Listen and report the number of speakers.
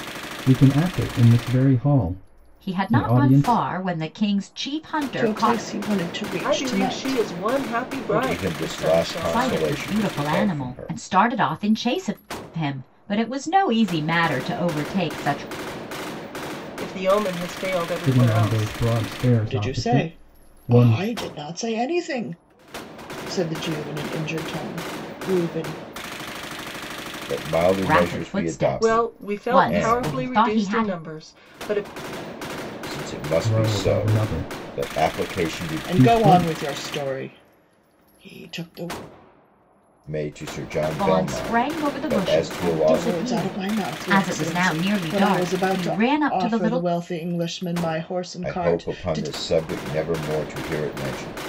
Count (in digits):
5